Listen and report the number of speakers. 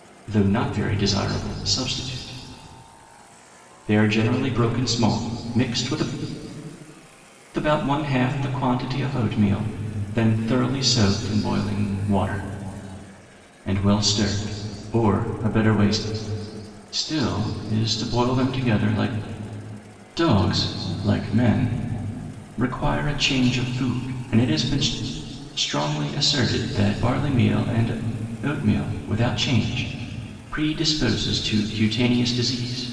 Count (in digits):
1